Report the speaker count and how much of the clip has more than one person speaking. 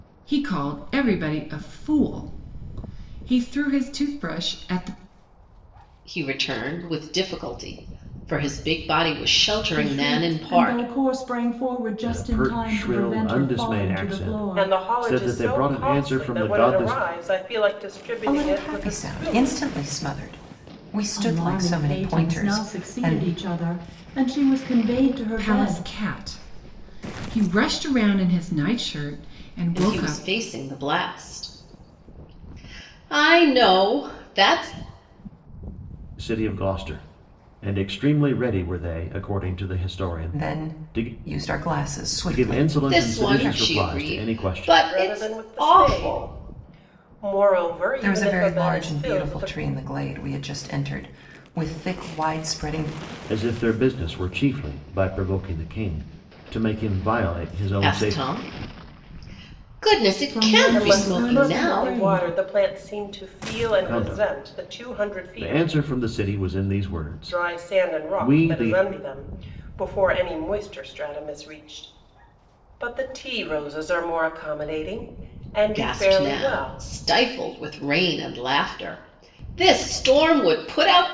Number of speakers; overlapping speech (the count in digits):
6, about 30%